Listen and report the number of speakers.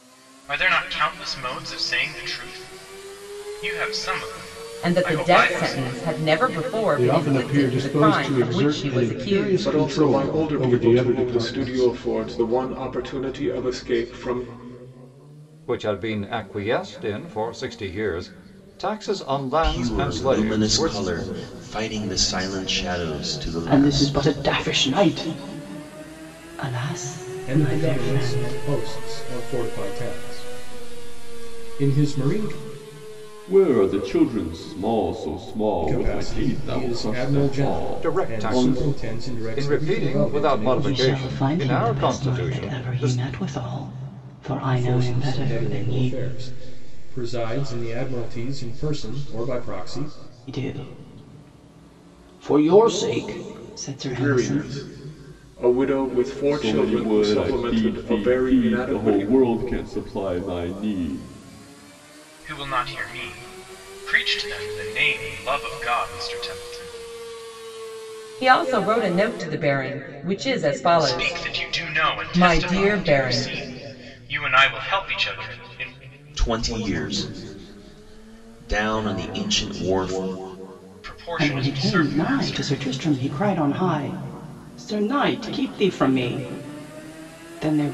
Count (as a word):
nine